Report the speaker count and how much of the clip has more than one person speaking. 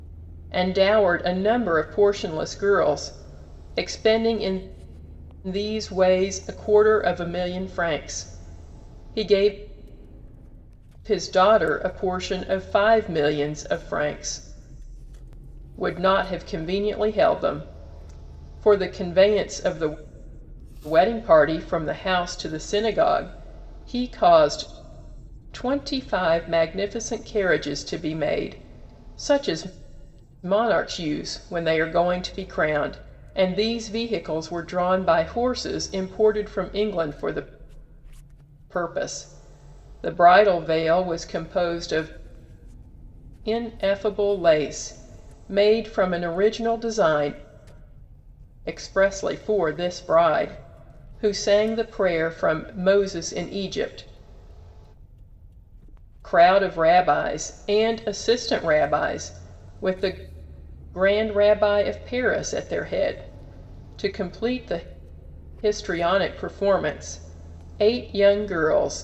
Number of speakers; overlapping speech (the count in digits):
1, no overlap